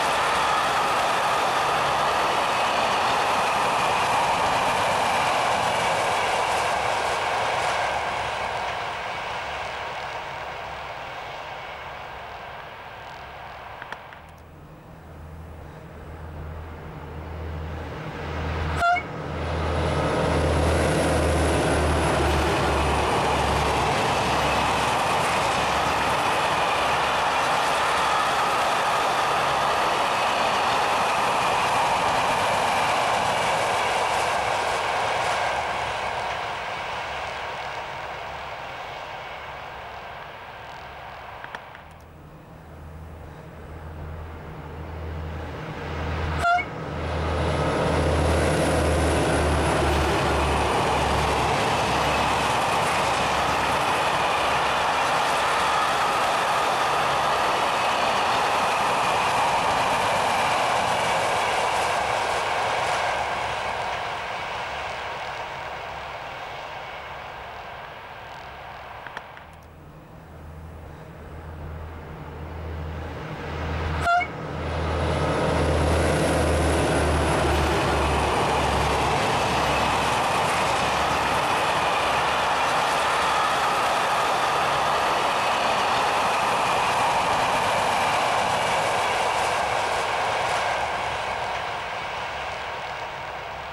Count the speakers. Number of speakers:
0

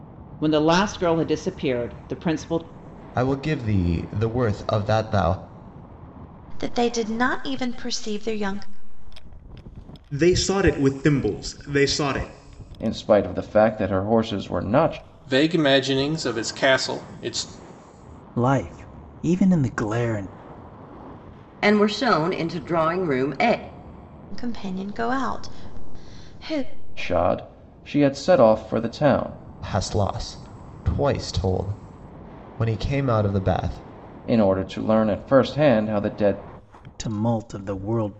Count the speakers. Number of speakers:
8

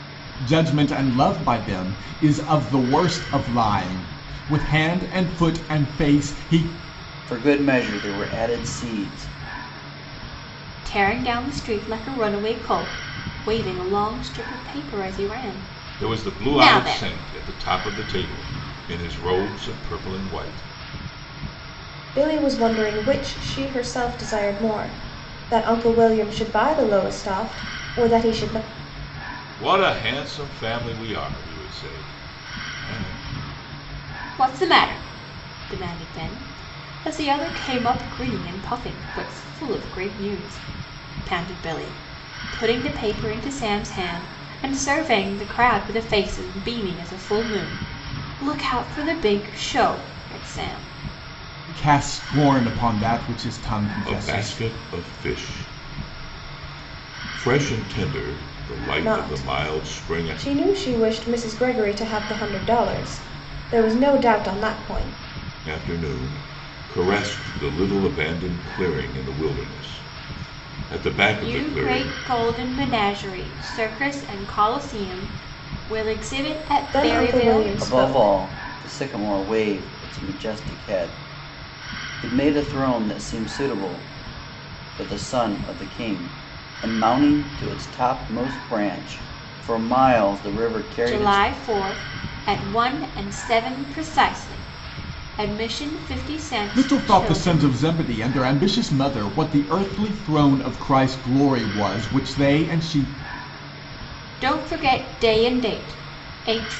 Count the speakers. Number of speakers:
5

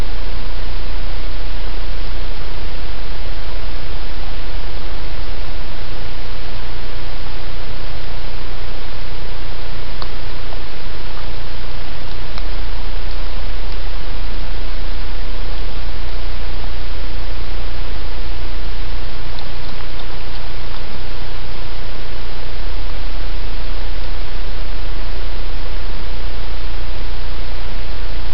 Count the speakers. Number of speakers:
0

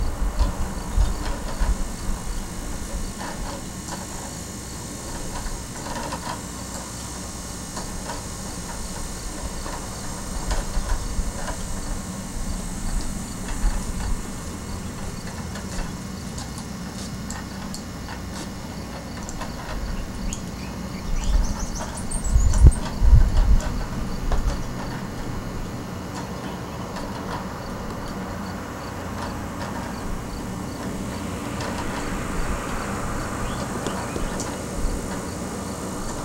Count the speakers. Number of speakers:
0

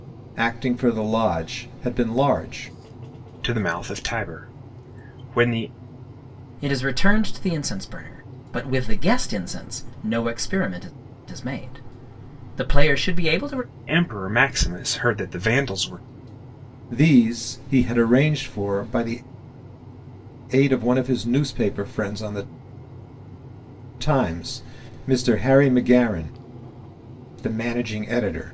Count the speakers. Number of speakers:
3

